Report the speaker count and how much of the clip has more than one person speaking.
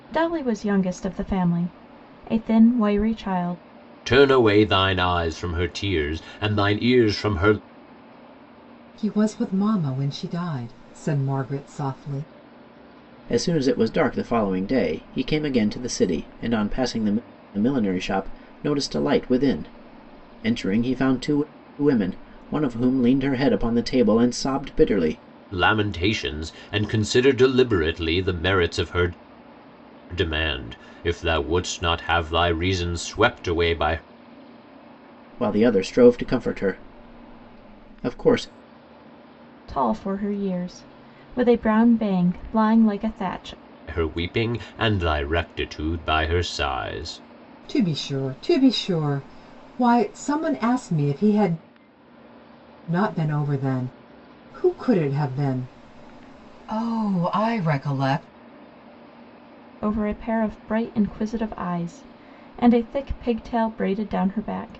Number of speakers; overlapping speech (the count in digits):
4, no overlap